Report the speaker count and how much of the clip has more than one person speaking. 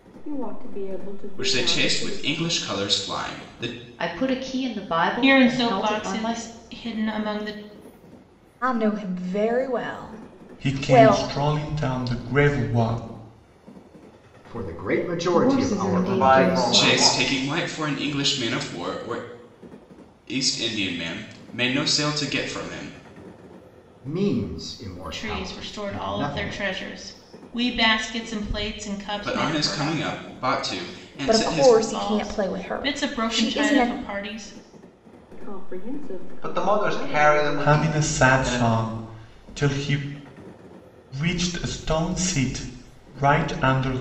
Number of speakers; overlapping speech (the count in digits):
9, about 28%